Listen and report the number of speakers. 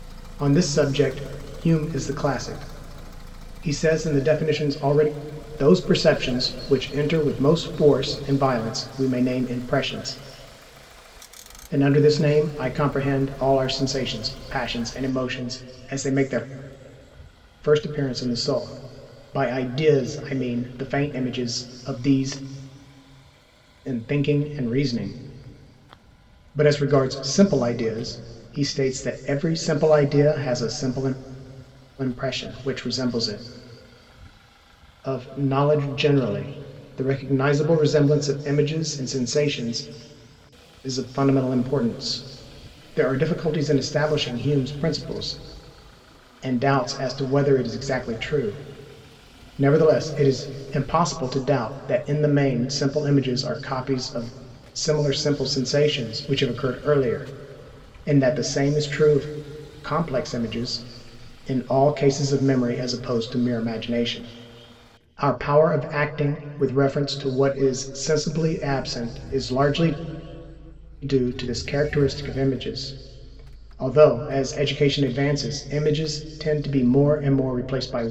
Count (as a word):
one